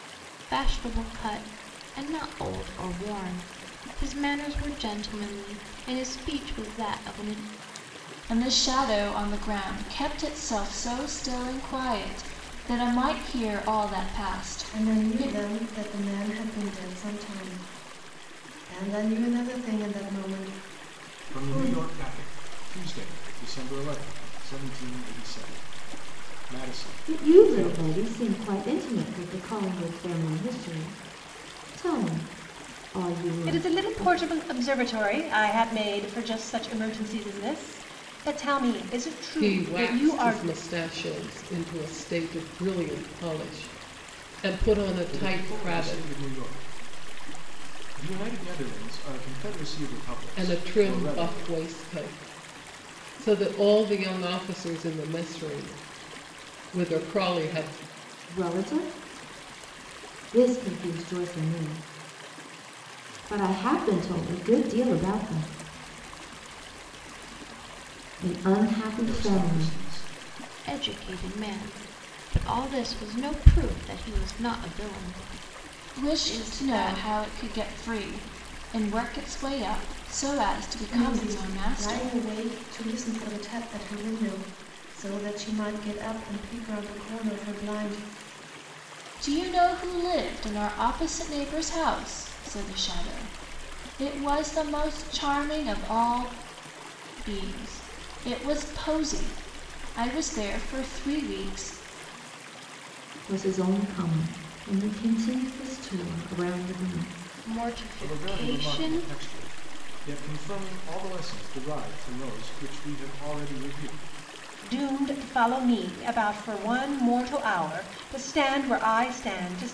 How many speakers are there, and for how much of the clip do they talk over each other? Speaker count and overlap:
seven, about 9%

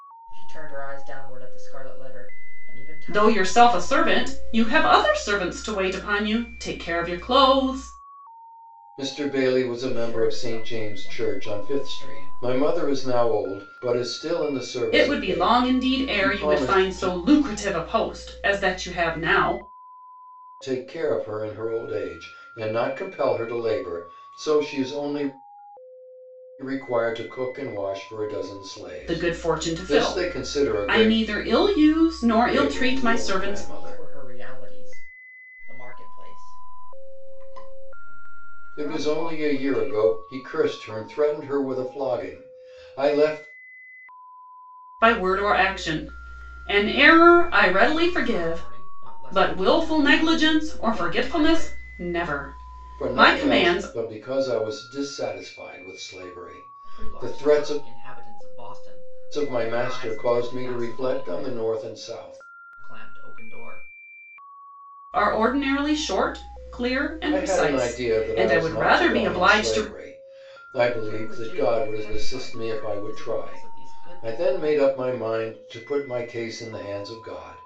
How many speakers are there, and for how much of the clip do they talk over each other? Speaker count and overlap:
three, about 36%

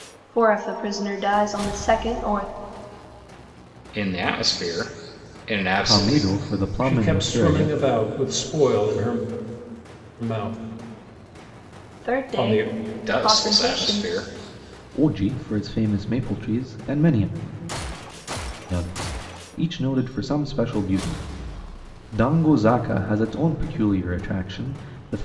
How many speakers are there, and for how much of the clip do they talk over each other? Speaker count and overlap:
four, about 13%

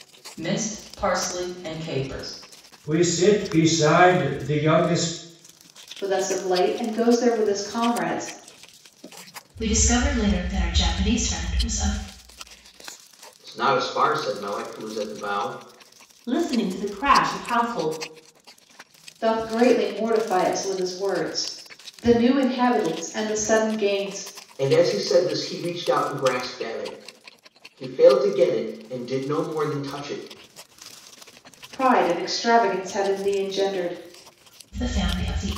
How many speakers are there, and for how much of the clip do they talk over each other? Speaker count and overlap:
six, no overlap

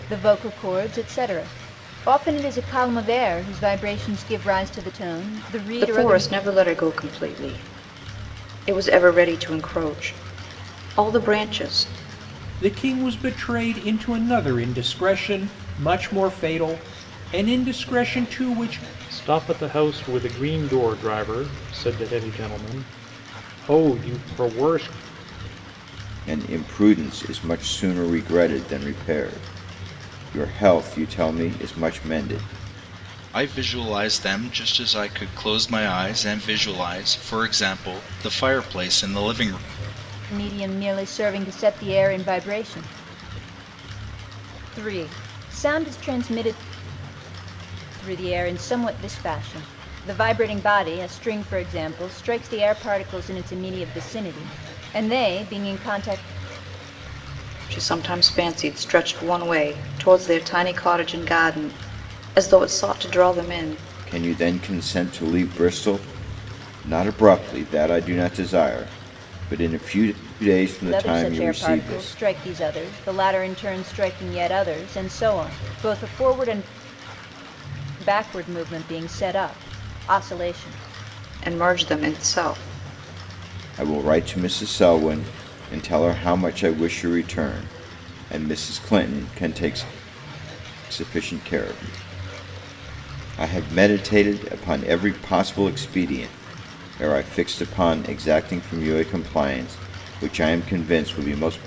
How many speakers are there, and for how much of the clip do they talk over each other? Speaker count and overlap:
six, about 2%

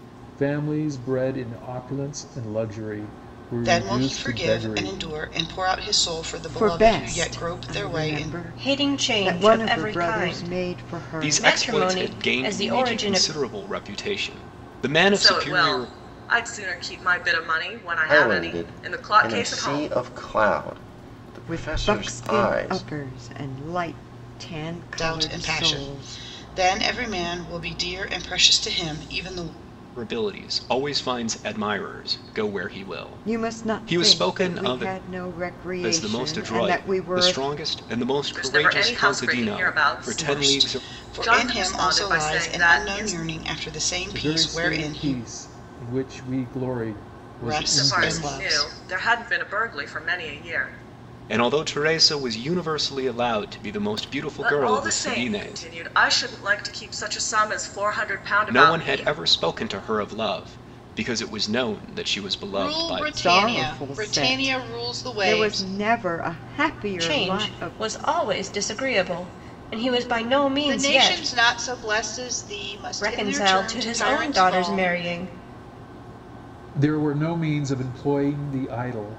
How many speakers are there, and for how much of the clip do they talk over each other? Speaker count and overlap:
seven, about 42%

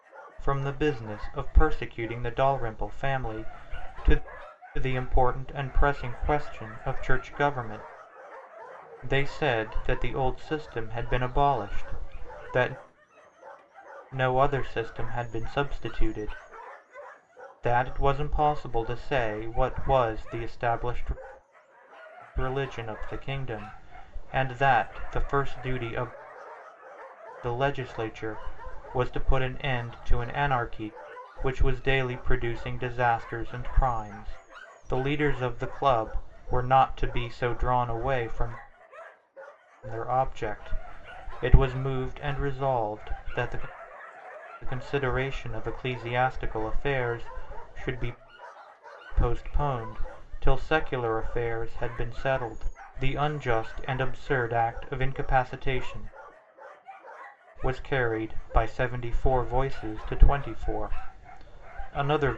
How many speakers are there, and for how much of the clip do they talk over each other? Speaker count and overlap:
one, no overlap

